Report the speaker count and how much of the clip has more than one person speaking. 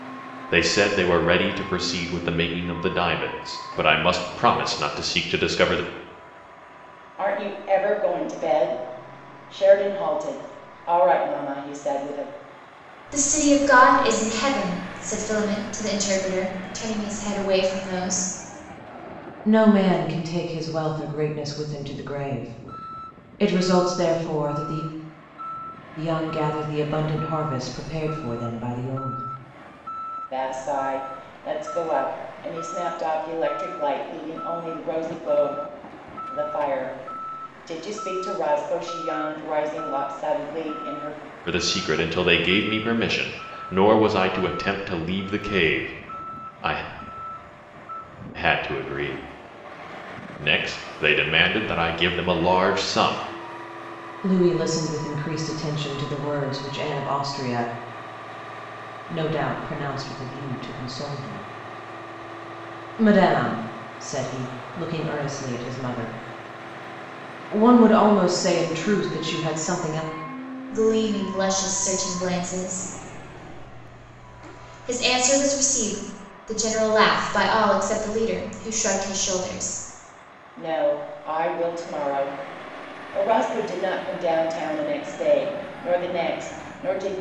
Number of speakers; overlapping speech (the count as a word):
four, no overlap